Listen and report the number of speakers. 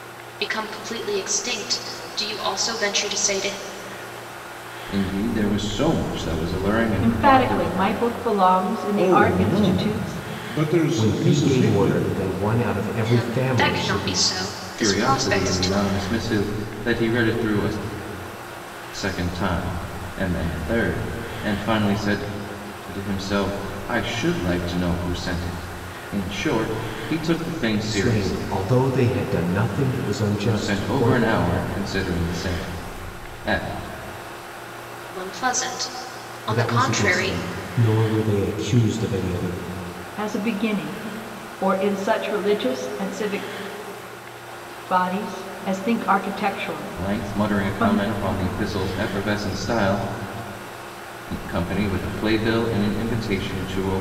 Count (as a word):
five